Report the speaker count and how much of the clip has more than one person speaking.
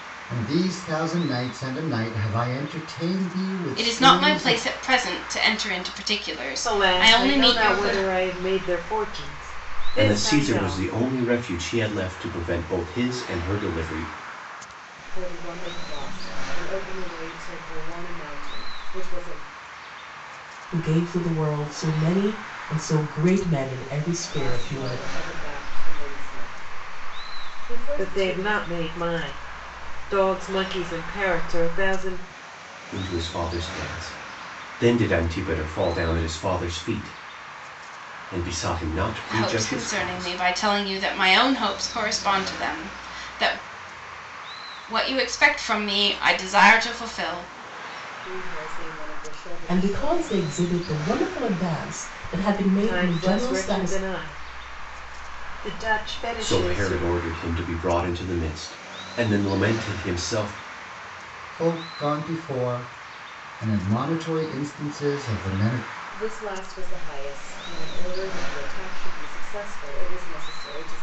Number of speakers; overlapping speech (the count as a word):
six, about 12%